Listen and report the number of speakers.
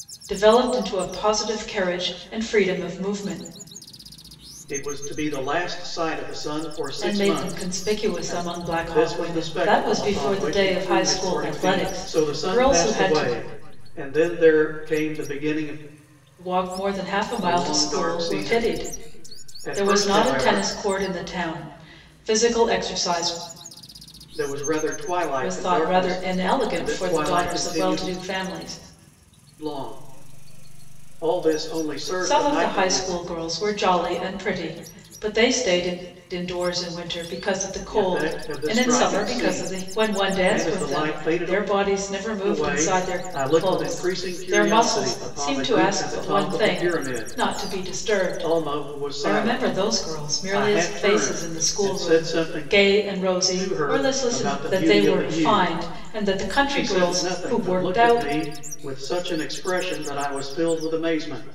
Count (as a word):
two